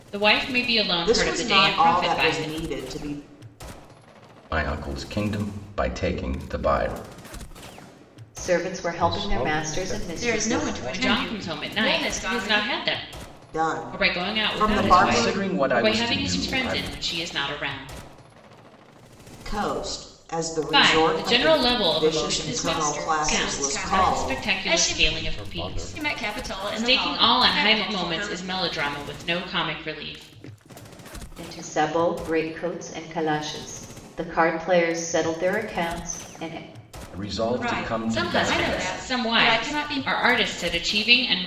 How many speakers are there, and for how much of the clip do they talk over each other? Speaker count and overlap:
6, about 44%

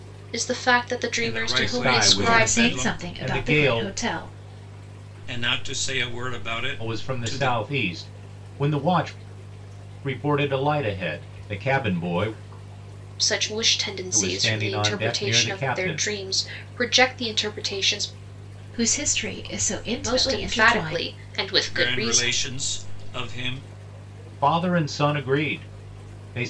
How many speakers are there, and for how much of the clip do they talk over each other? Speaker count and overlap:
4, about 28%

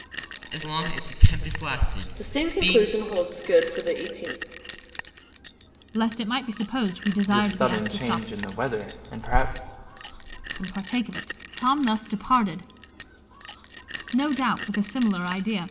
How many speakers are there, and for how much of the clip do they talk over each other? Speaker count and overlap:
4, about 12%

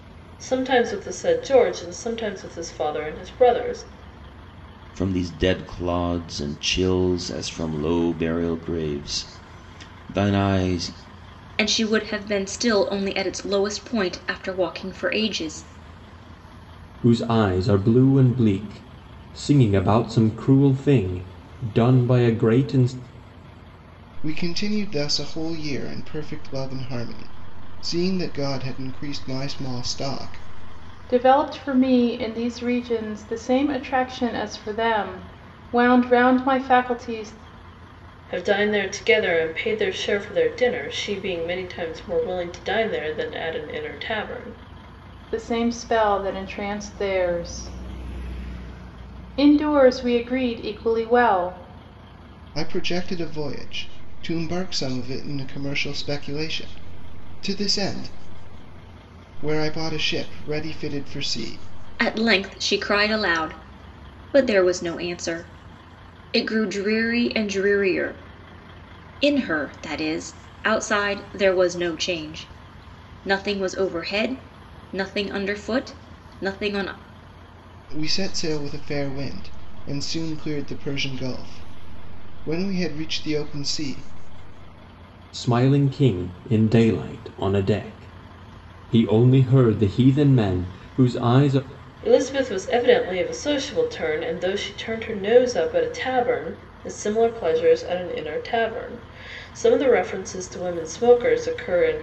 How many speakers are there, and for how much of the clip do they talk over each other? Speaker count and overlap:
6, no overlap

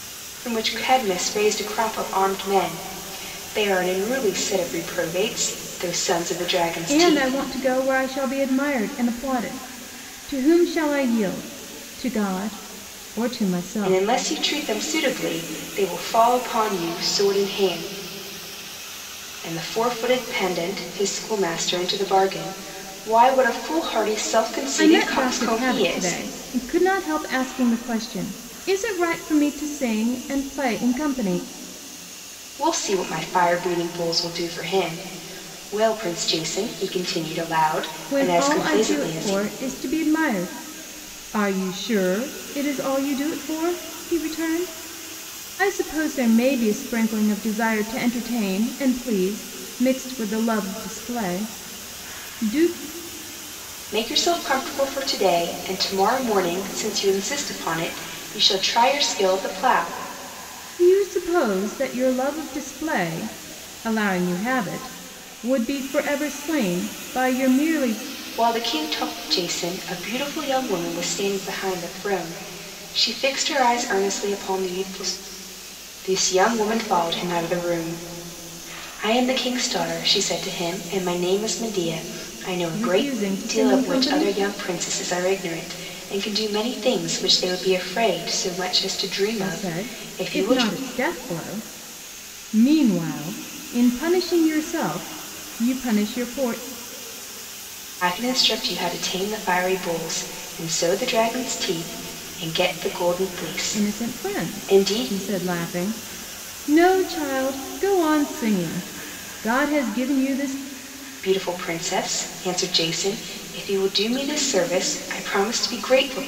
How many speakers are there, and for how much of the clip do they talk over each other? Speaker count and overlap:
2, about 7%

